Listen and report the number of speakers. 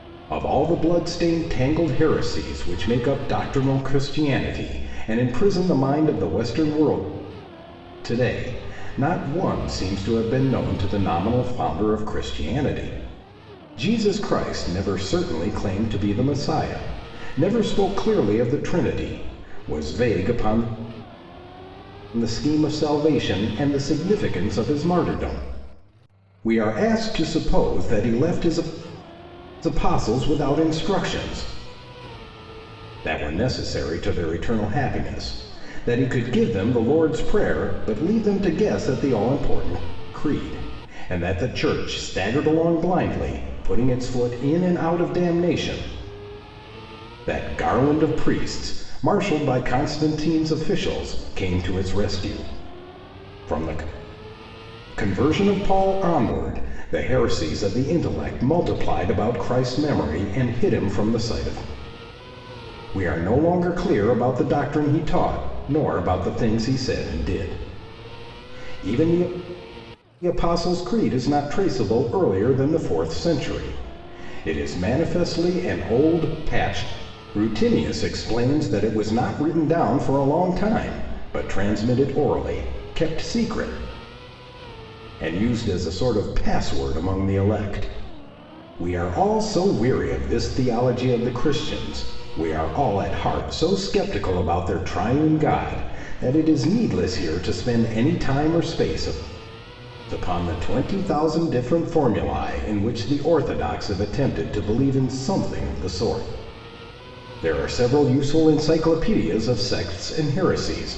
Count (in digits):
1